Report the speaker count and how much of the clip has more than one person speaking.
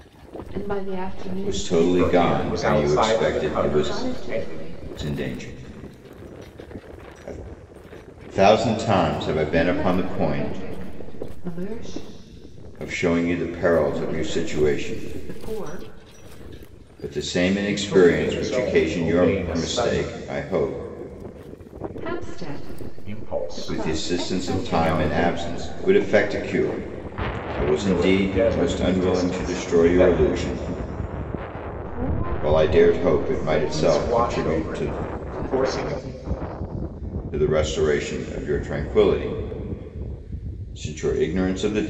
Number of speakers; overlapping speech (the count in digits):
3, about 40%